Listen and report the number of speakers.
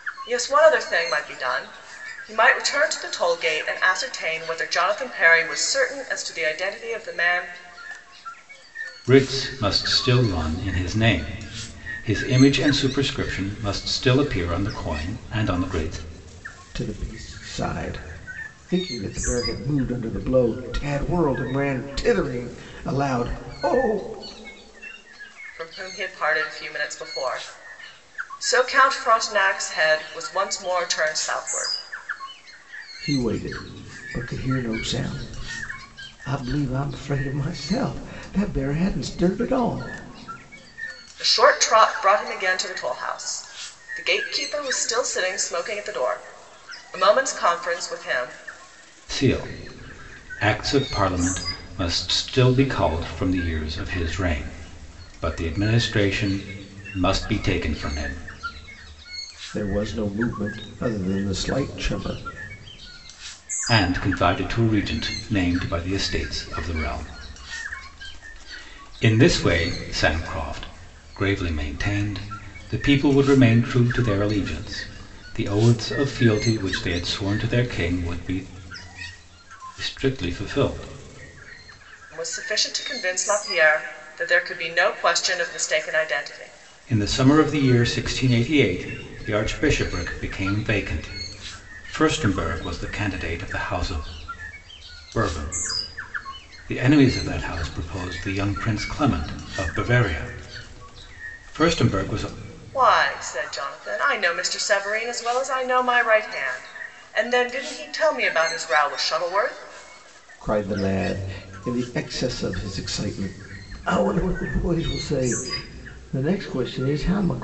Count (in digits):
3